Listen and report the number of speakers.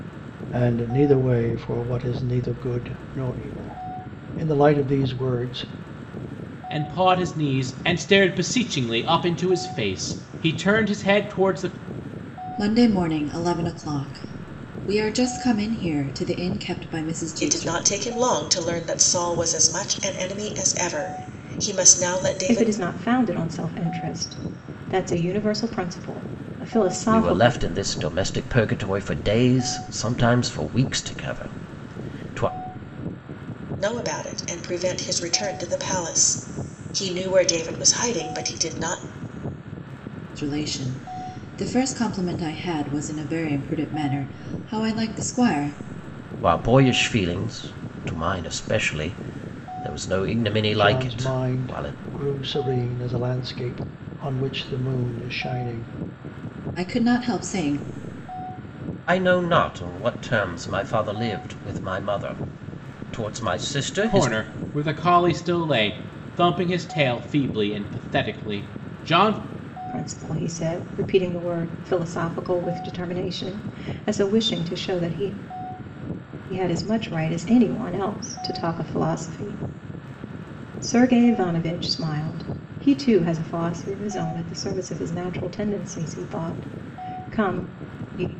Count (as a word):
six